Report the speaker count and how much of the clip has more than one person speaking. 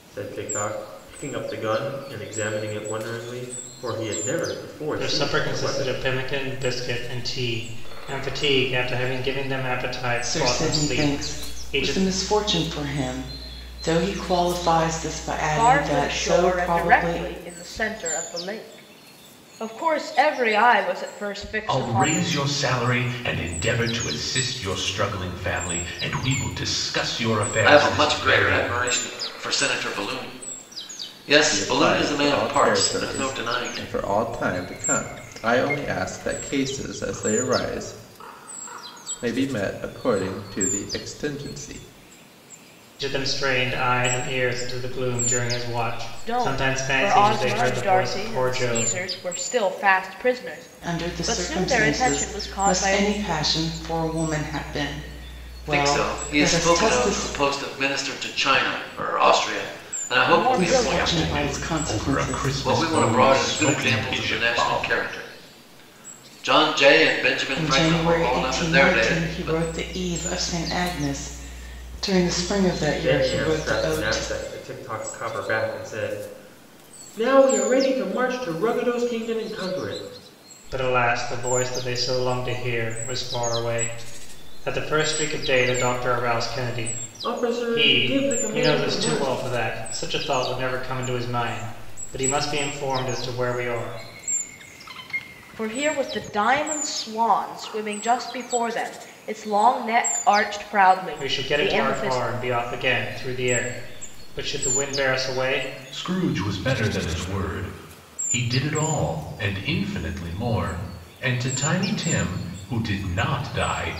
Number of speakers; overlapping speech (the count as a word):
seven, about 24%